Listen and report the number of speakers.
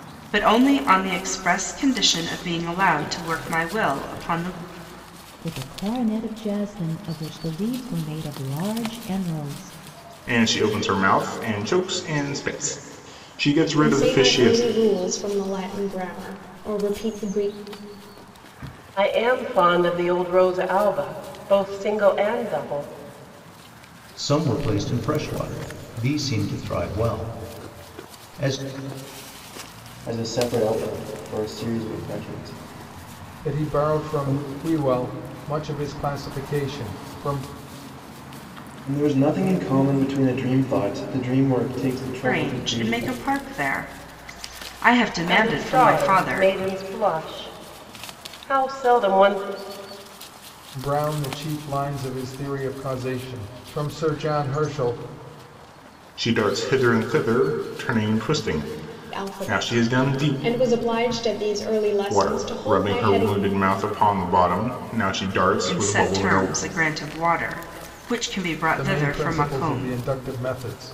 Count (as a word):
eight